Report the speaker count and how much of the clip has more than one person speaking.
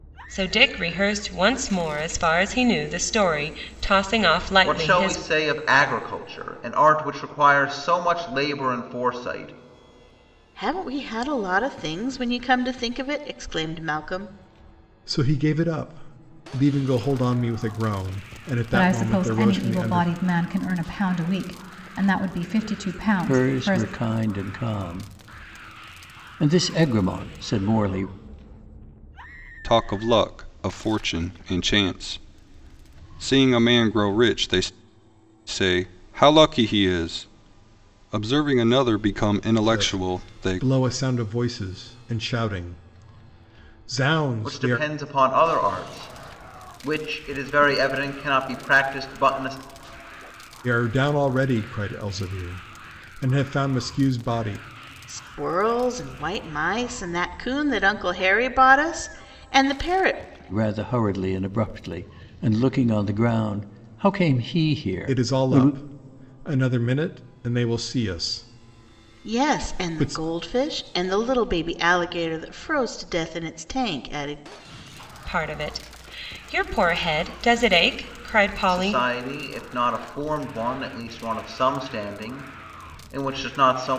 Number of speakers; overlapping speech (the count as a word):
seven, about 8%